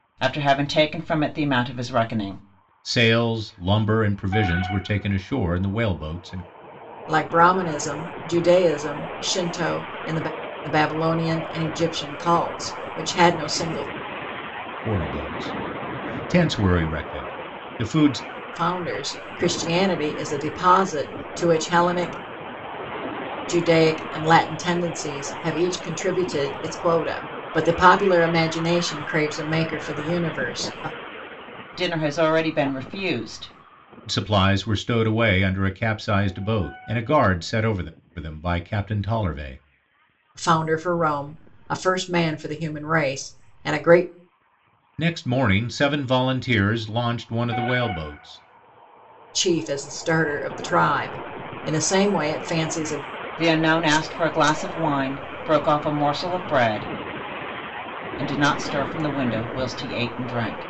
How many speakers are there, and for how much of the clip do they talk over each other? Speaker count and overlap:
three, no overlap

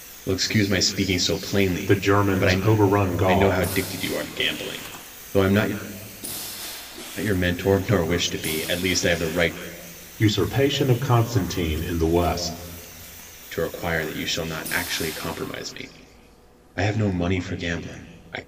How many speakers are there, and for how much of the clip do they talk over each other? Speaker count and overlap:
two, about 6%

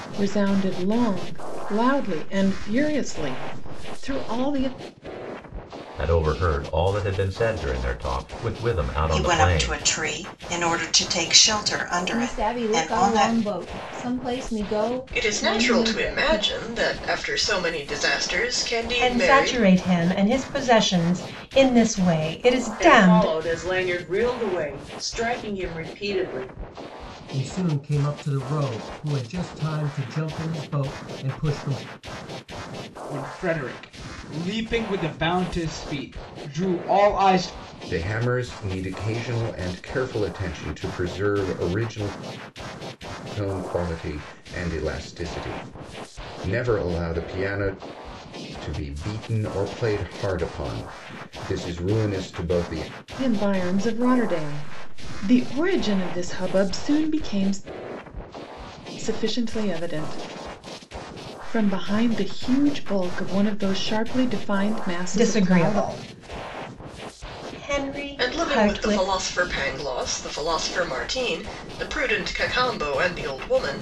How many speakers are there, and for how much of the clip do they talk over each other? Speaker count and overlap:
ten, about 9%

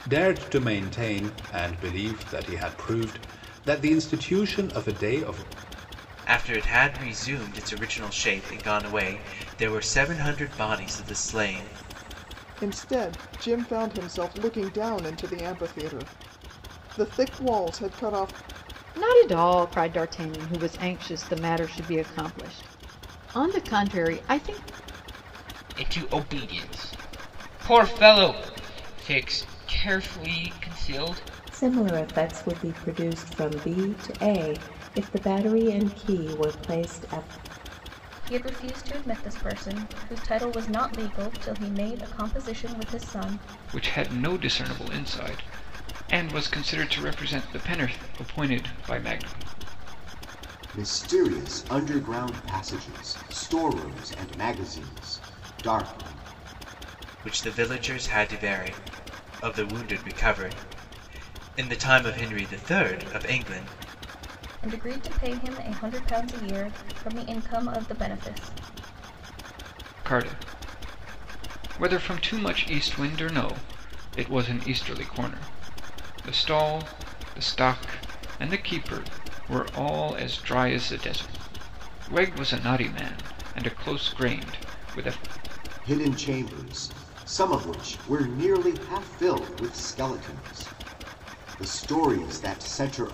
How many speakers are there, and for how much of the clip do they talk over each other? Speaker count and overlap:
nine, no overlap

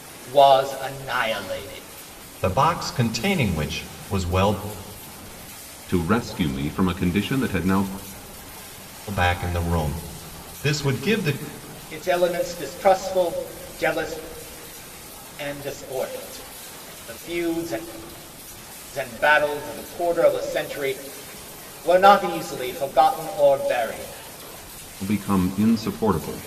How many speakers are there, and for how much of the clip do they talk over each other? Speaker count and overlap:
three, no overlap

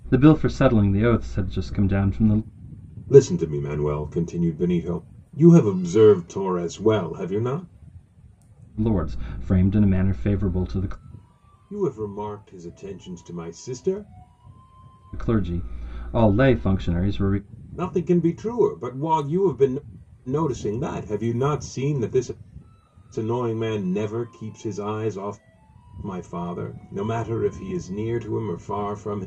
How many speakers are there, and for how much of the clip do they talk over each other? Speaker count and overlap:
two, no overlap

